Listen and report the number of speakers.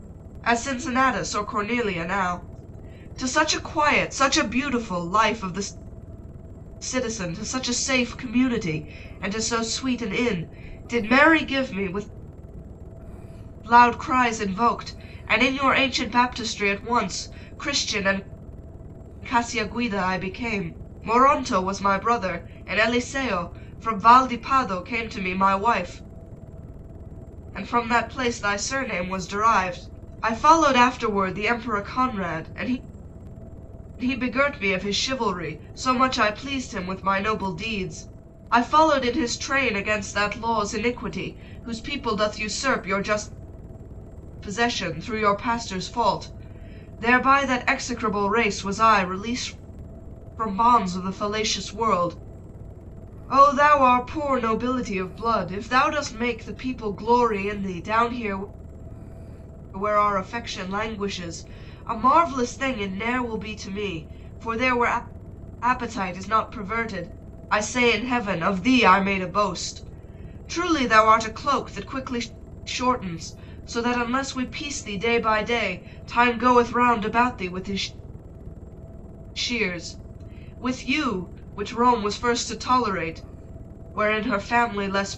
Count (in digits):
1